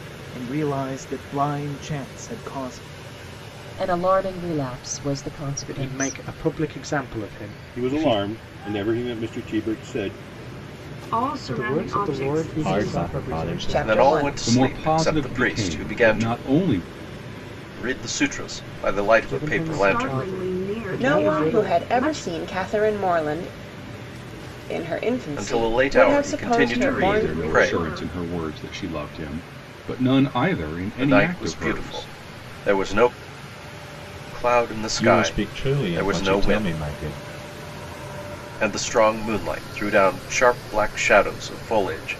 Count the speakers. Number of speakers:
ten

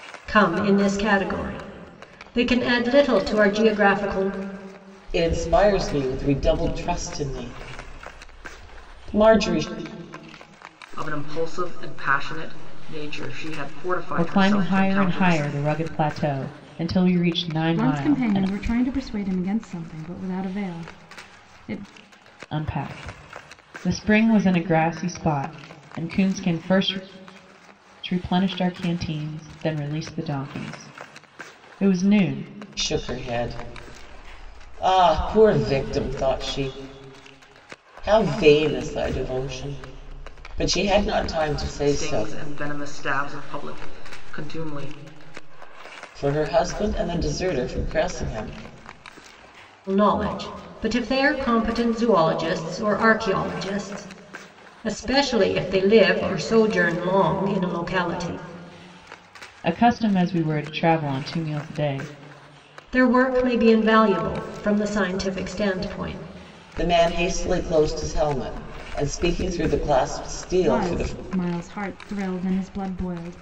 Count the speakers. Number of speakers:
five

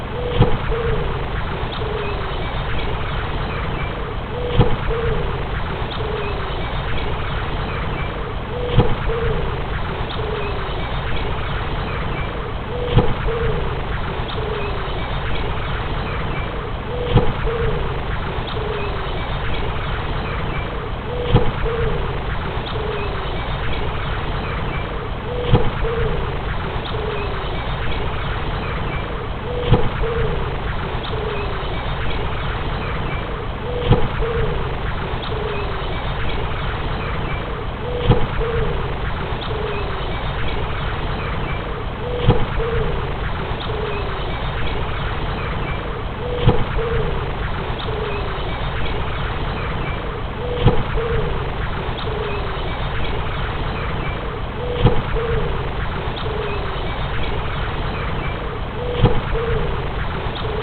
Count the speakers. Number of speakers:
zero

